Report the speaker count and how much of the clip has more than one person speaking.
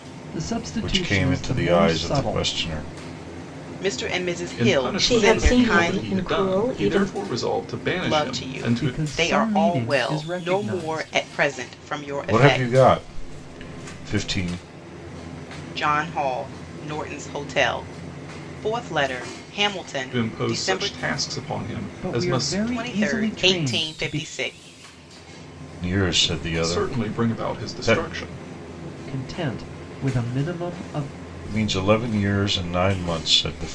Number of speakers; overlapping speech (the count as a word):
five, about 37%